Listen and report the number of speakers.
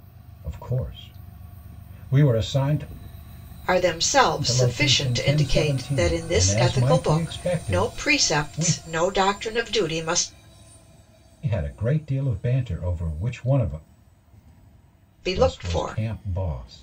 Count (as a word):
two